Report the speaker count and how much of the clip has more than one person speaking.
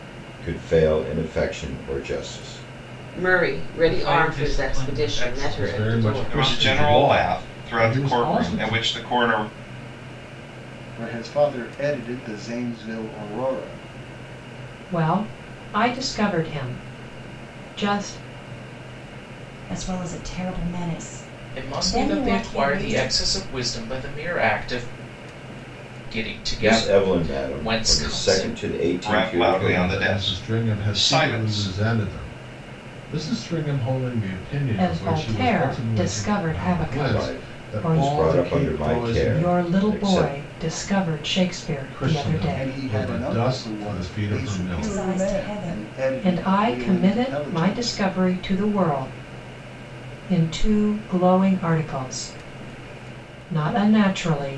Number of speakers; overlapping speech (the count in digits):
9, about 42%